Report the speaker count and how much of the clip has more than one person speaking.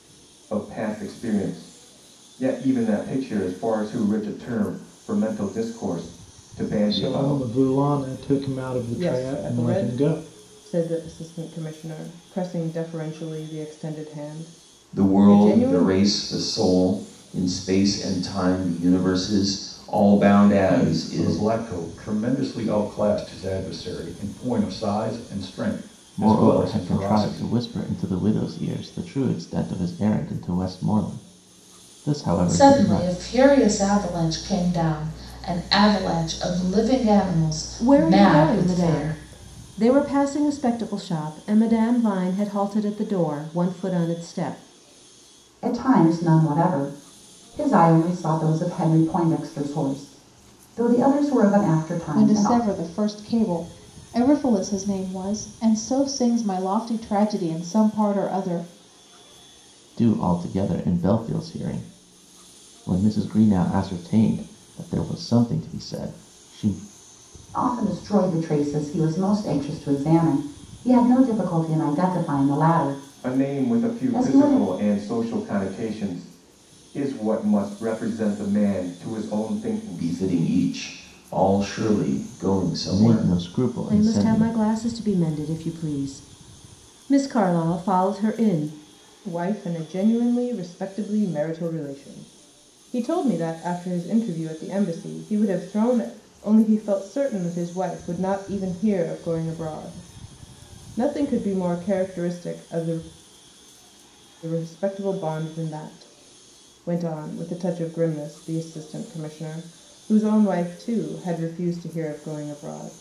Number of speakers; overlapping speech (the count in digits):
10, about 9%